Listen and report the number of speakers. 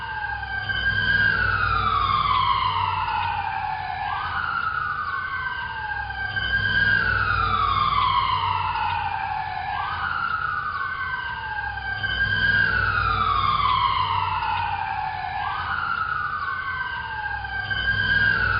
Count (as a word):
zero